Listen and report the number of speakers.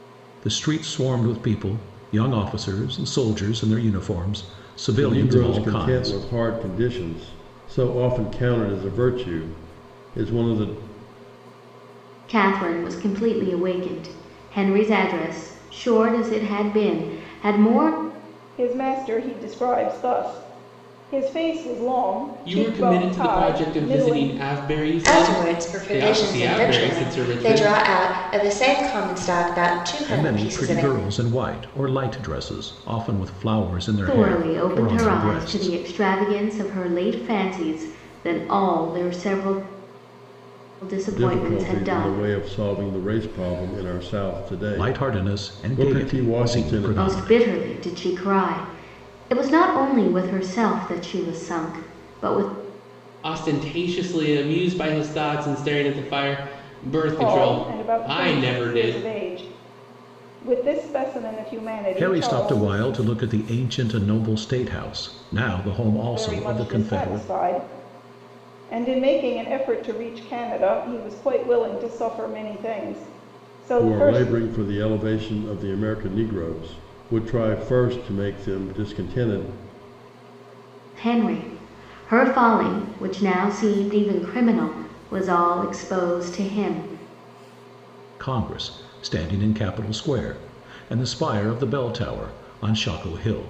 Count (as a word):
six